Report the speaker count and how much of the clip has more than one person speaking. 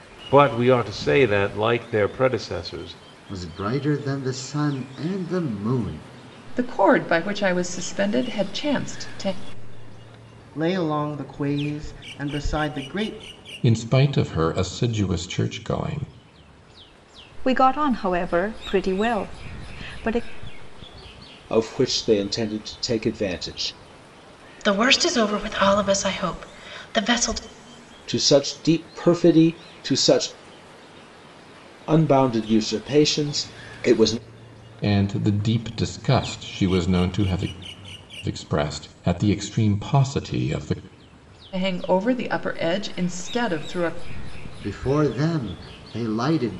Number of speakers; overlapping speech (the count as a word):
eight, no overlap